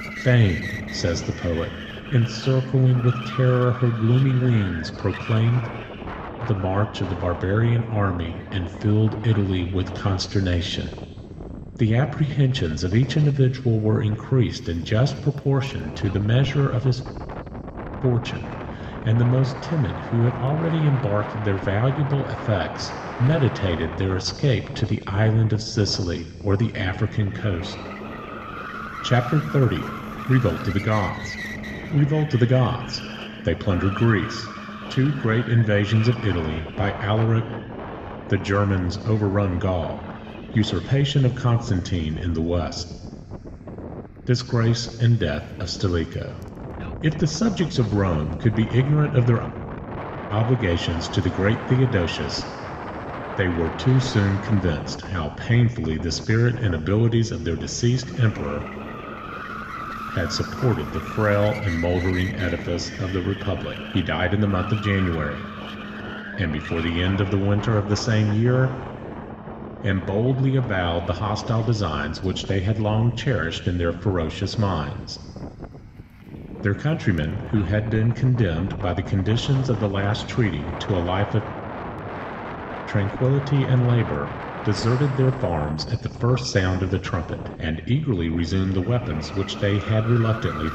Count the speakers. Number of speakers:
1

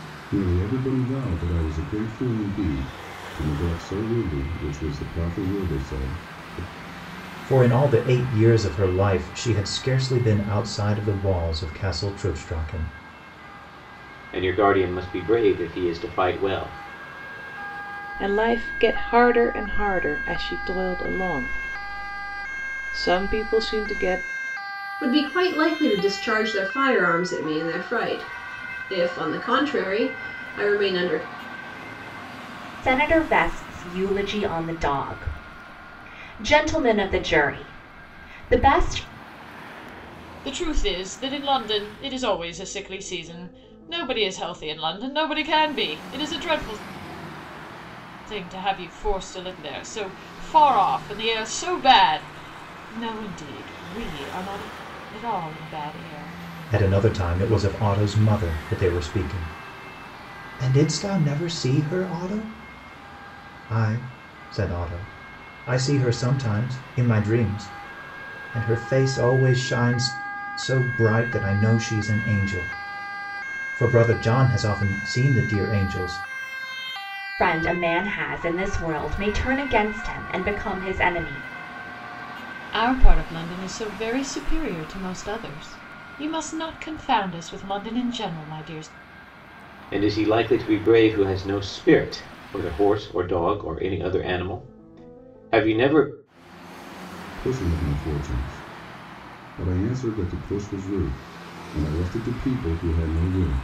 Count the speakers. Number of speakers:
7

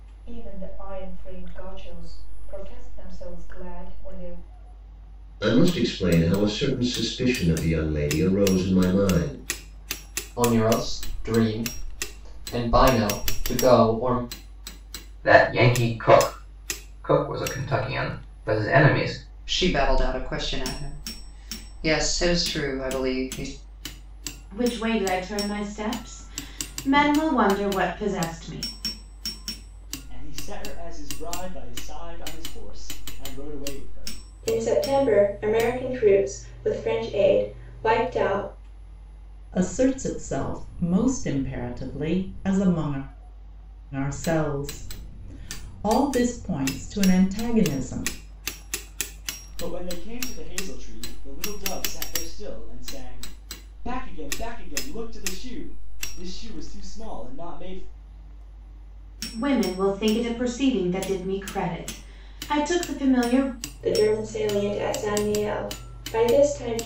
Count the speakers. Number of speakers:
9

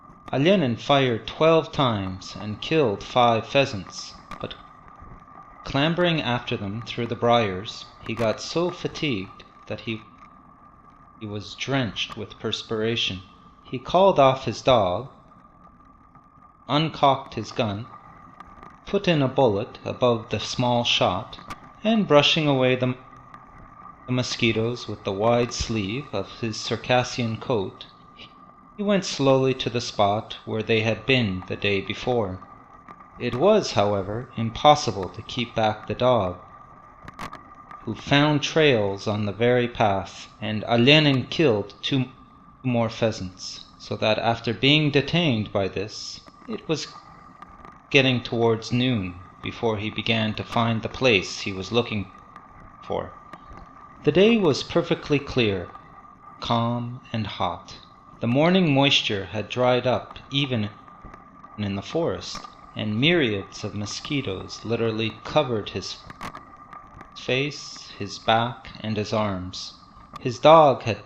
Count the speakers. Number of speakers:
1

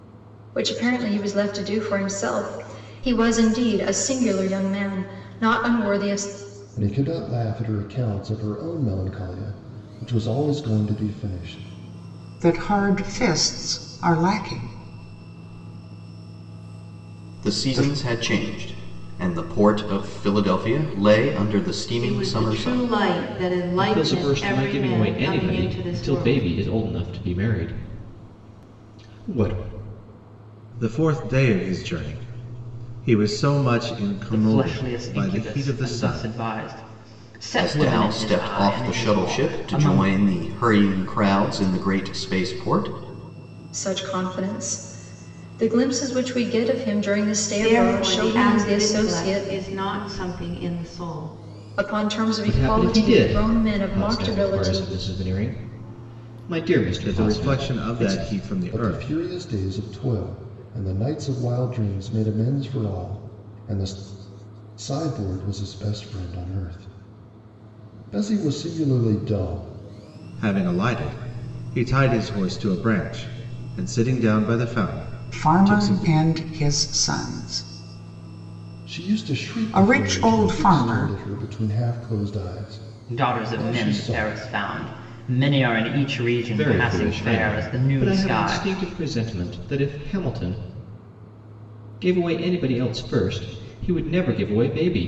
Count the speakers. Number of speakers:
8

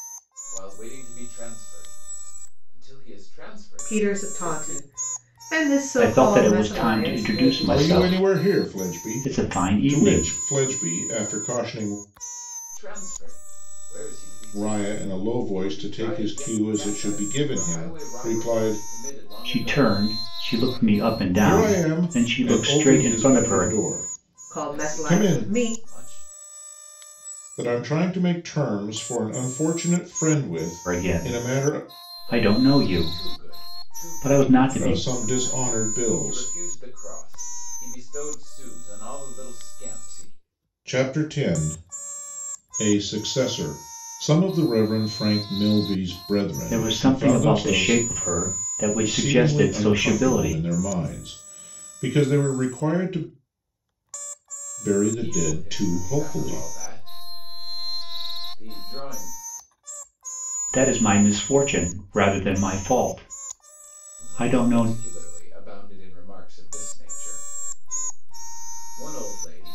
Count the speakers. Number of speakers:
4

